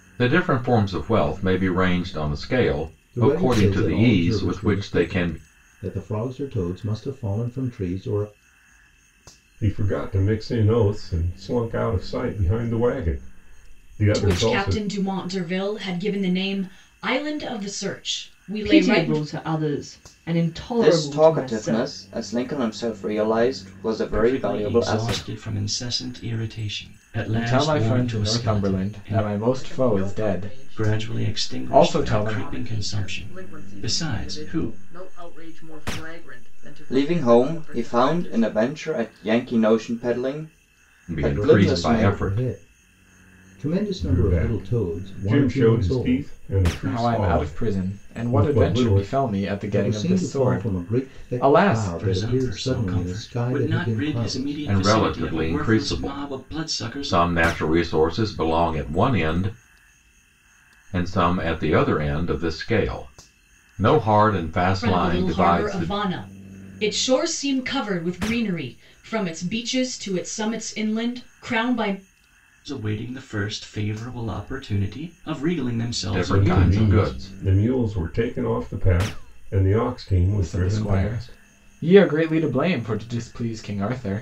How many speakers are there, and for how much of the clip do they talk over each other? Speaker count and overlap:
nine, about 38%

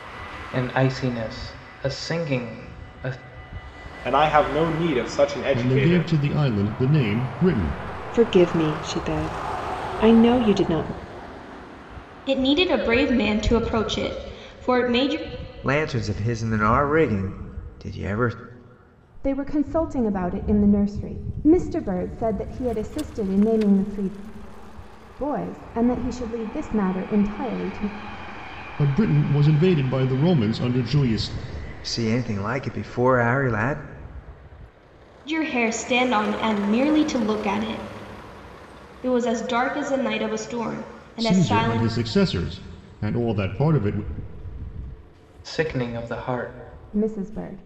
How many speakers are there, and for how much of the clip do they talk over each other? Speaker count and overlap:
seven, about 3%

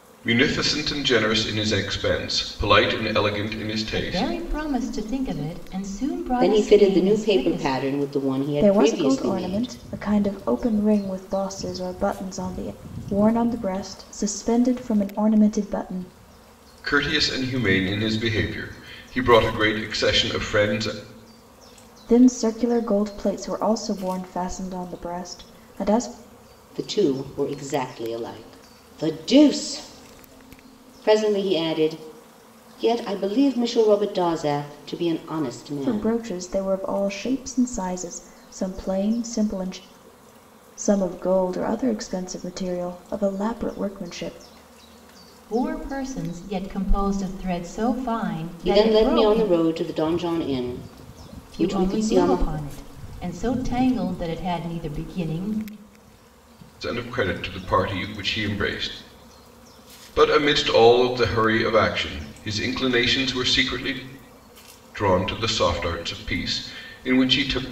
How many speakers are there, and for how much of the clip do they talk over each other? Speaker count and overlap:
four, about 8%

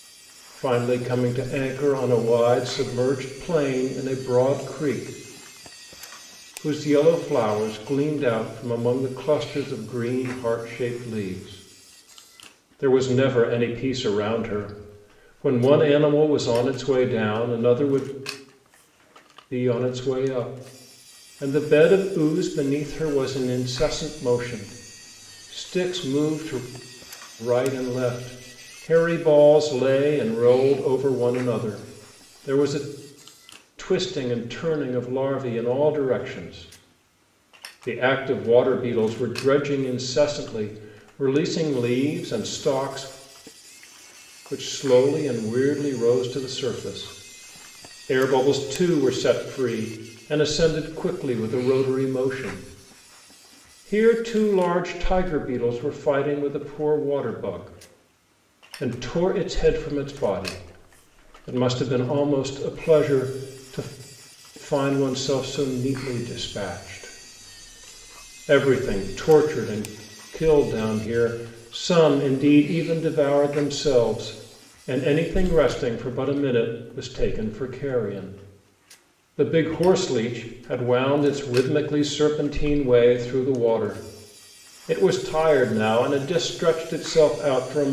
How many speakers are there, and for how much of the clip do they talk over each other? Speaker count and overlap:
one, no overlap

